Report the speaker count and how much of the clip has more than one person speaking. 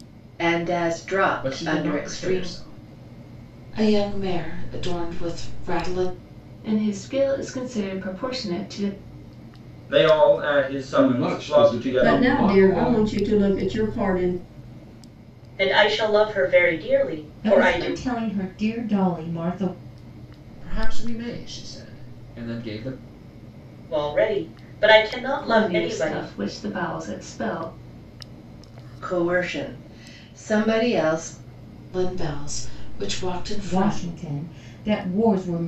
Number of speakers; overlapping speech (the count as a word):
nine, about 15%